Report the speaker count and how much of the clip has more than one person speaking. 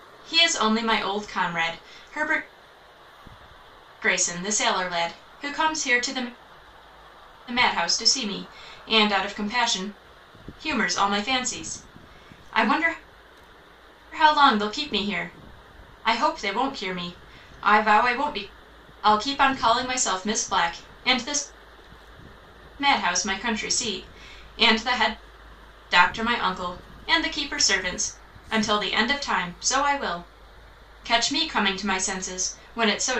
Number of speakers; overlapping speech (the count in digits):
1, no overlap